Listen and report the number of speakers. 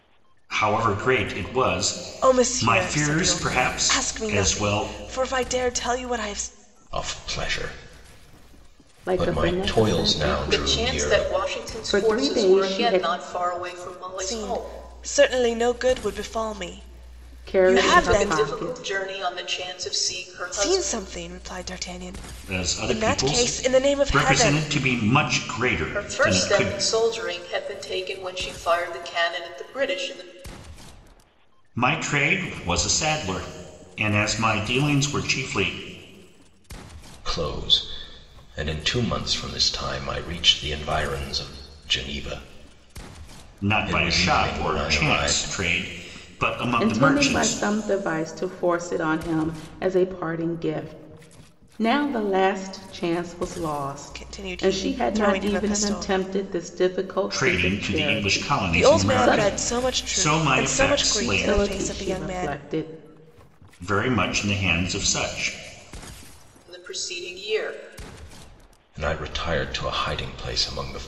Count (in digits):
5